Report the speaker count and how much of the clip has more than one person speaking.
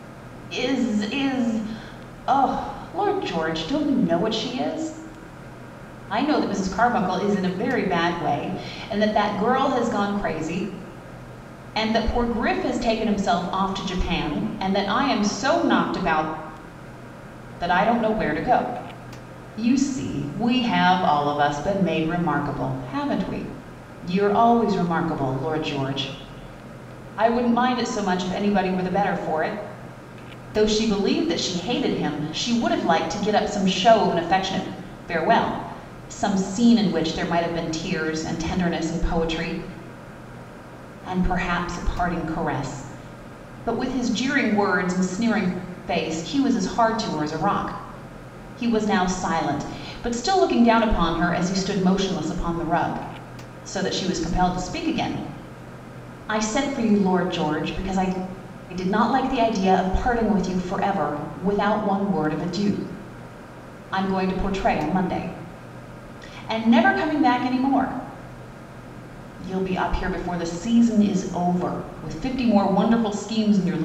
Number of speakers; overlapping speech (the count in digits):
1, no overlap